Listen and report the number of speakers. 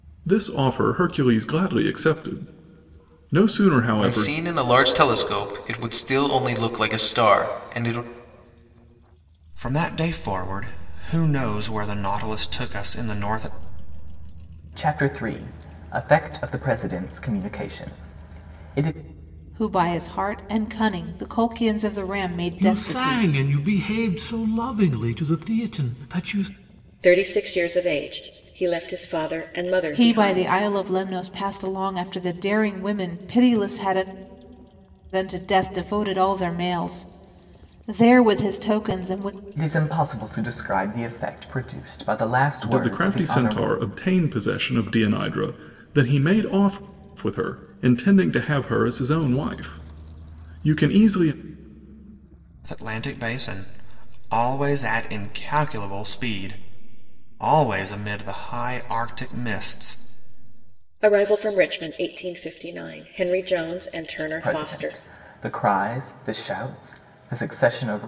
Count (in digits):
7